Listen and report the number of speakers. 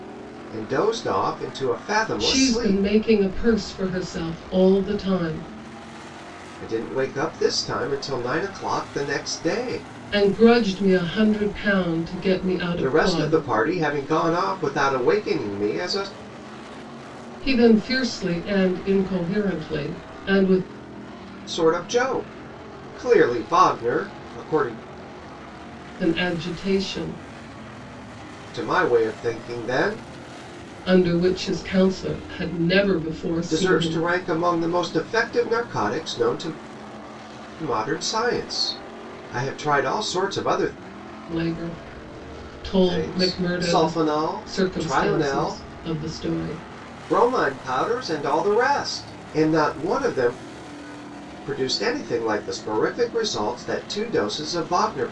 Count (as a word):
two